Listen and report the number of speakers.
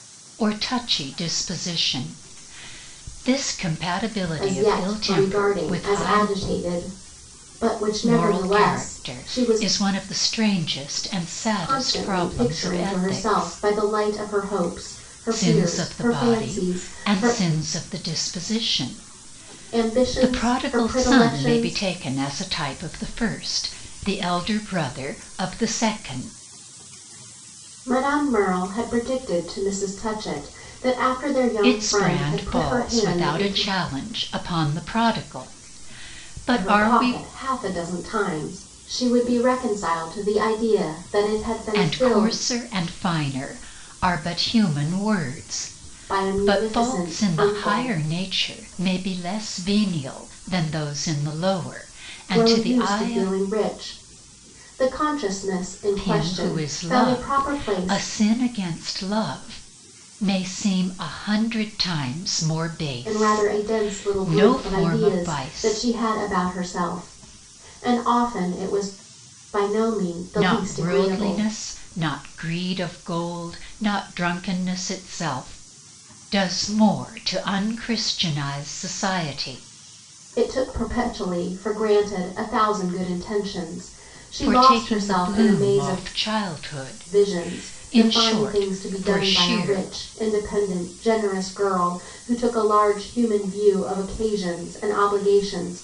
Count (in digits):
2